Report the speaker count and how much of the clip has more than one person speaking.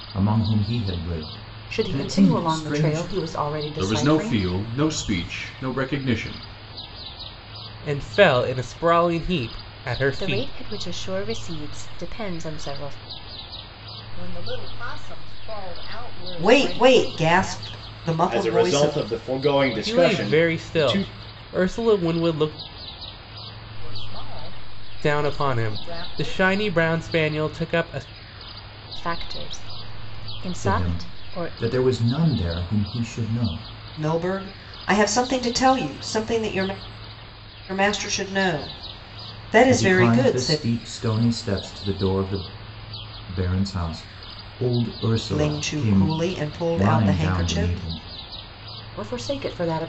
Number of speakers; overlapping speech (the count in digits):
8, about 22%